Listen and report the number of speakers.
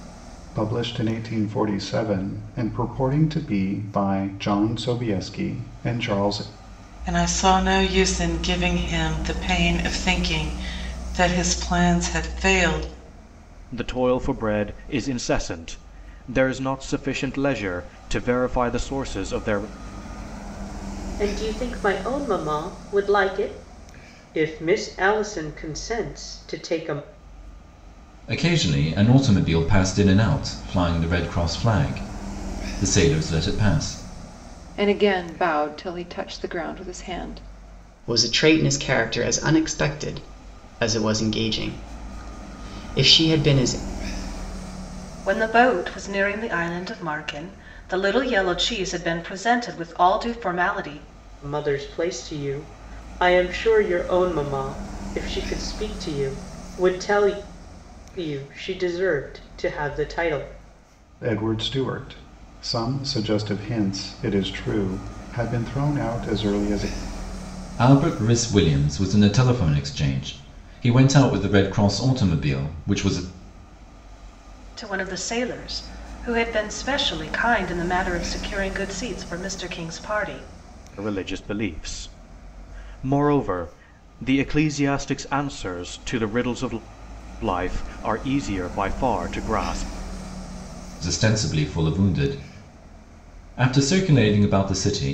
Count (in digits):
8